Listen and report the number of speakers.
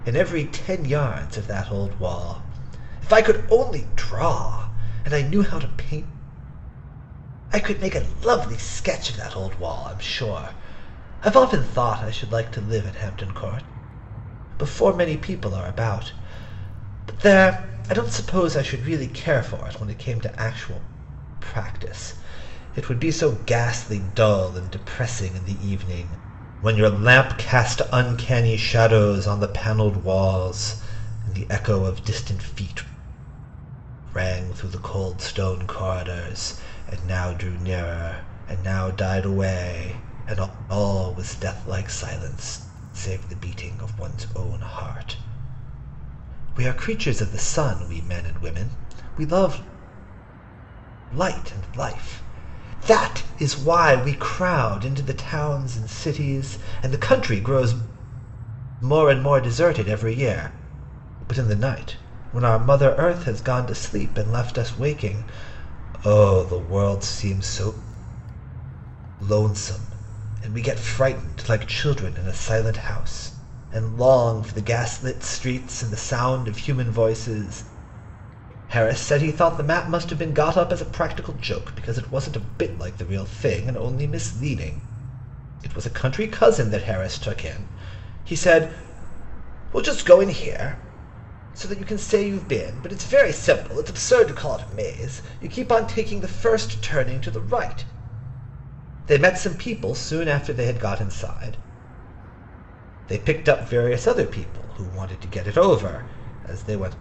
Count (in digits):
1